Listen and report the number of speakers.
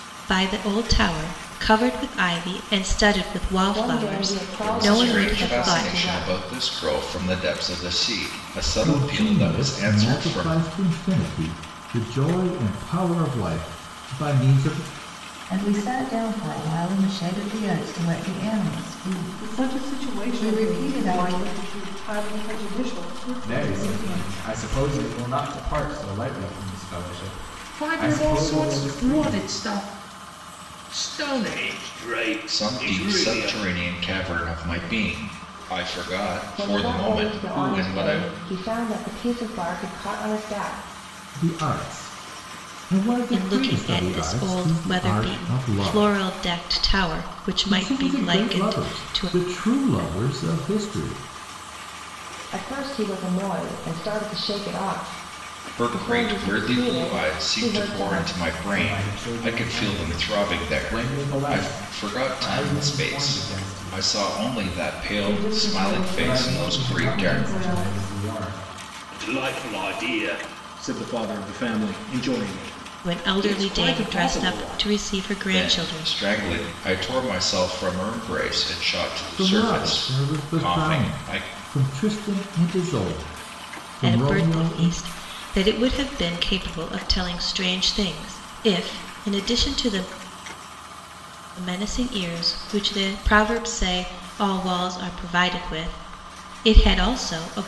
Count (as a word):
eight